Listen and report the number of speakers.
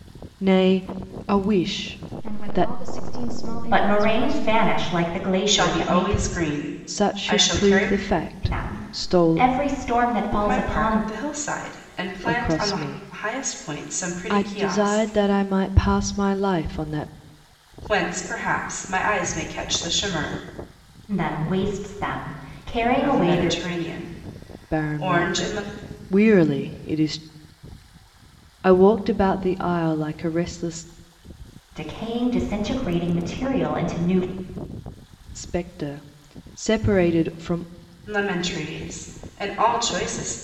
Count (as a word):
four